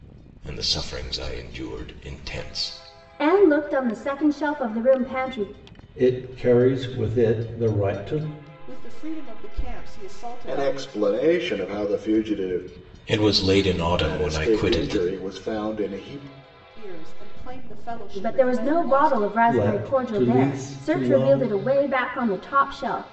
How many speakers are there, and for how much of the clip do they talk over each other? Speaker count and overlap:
5, about 19%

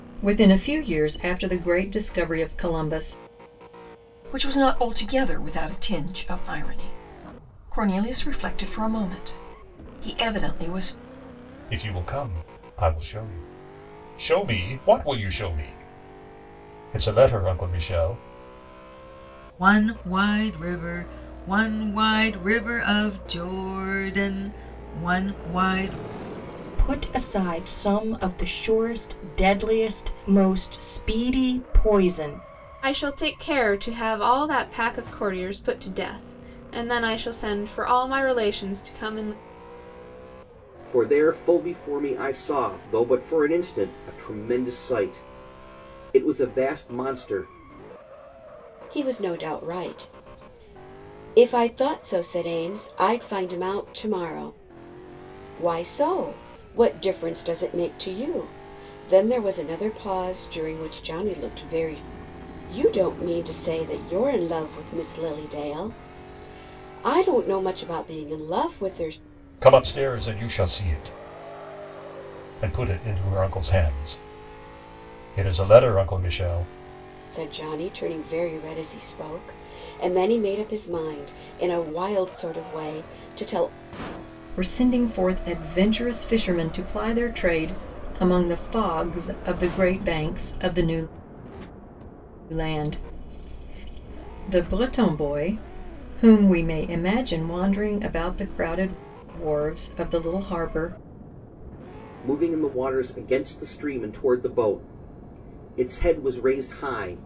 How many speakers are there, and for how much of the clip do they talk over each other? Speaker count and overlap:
8, no overlap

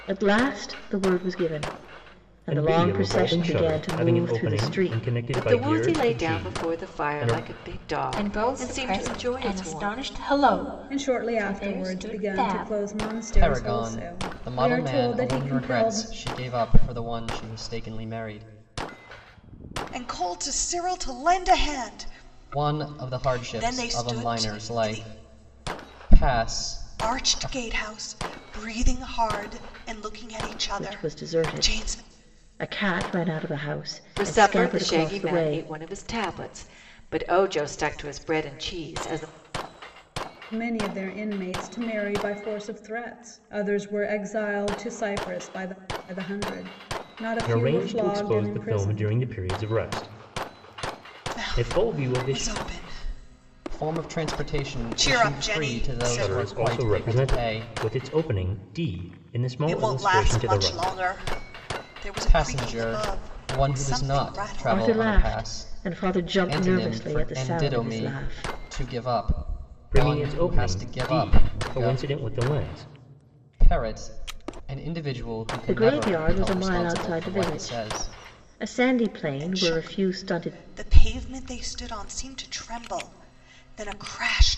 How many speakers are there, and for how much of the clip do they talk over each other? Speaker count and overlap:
7, about 45%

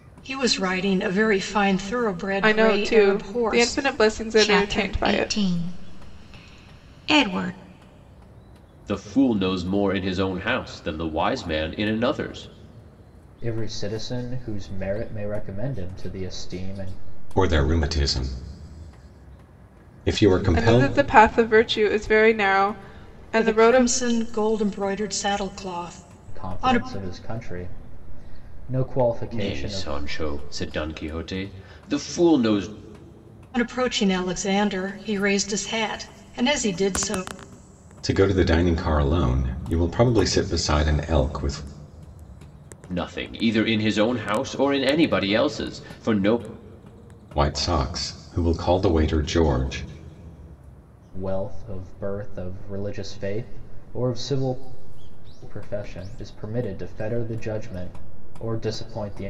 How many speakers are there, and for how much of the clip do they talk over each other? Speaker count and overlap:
6, about 8%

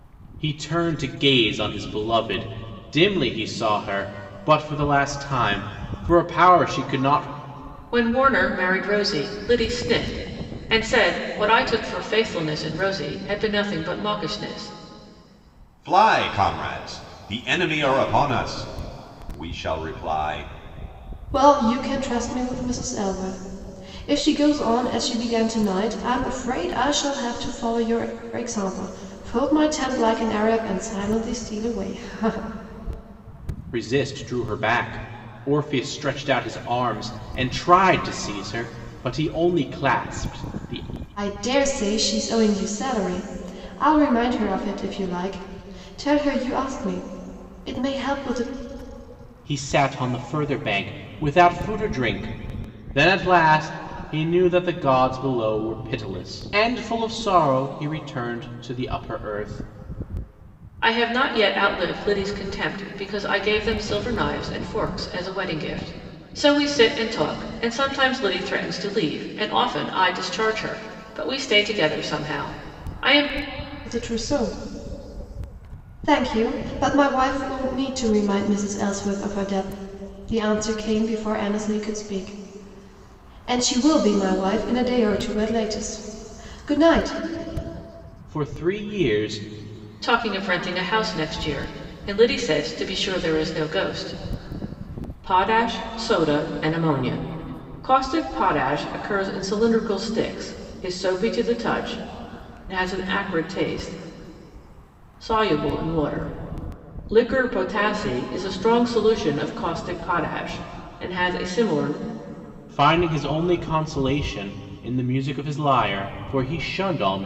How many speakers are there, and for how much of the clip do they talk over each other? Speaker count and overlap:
4, no overlap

